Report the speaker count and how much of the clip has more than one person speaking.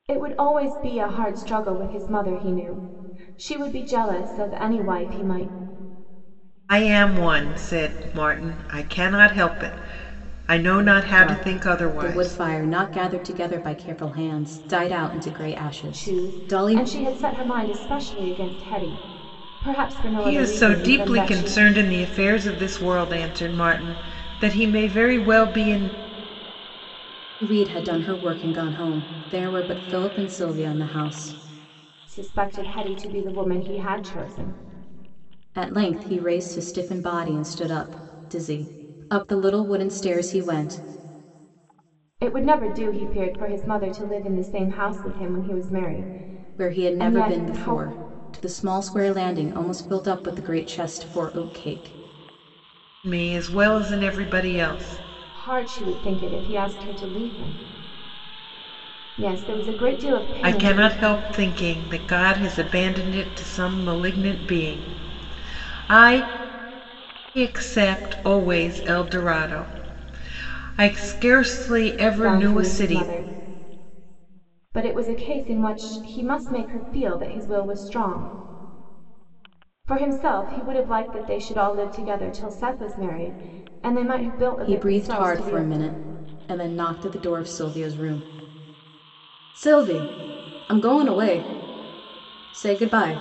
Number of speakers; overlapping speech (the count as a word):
three, about 8%